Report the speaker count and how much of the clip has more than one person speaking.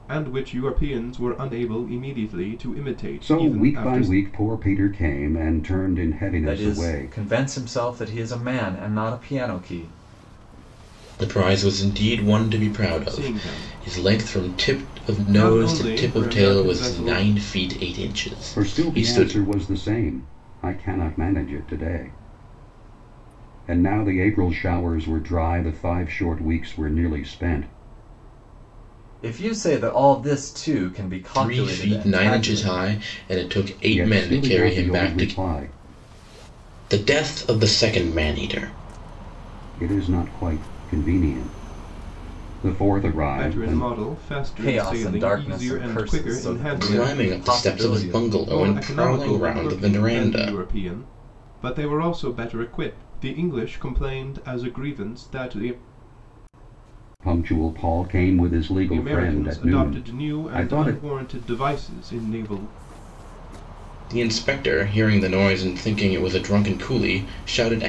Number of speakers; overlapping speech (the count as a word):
four, about 27%